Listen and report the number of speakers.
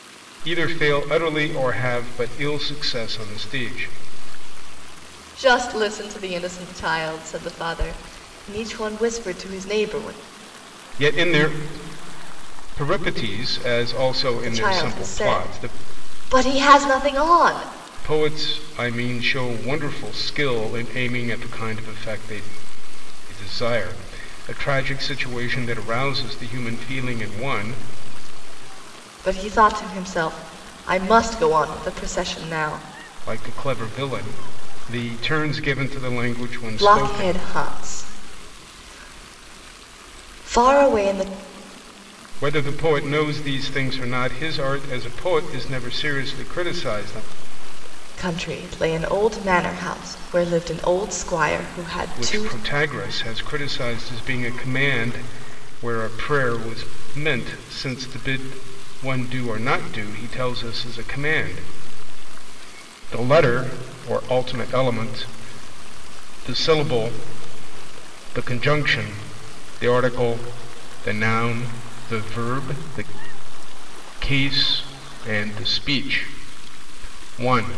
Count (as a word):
two